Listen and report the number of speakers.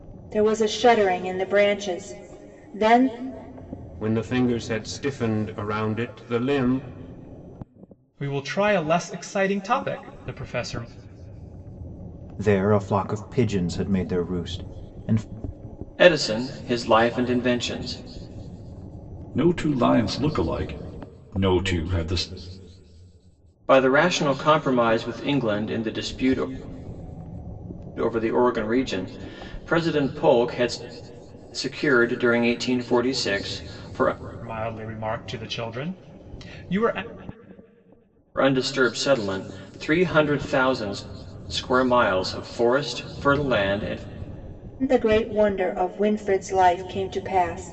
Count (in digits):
6